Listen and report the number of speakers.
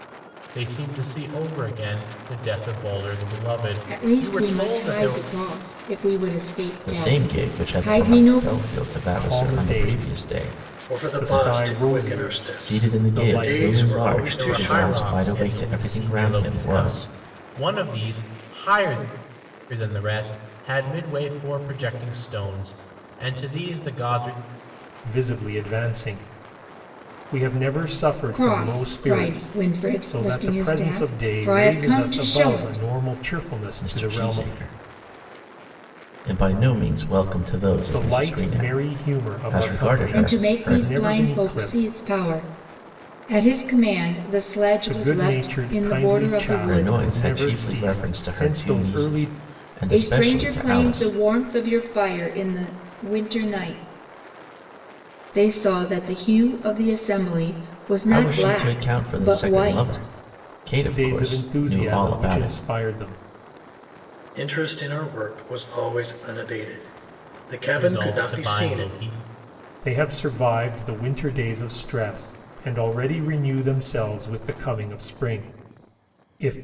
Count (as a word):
five